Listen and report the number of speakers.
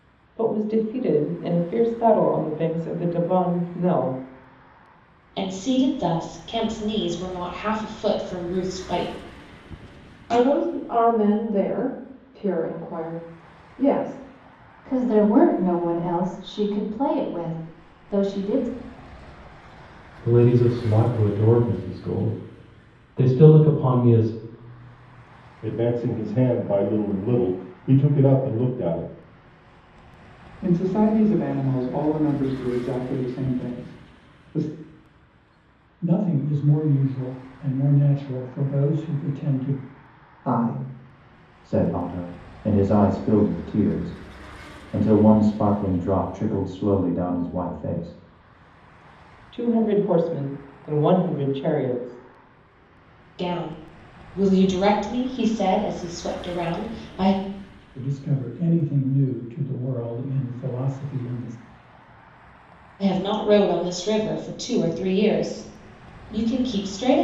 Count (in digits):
9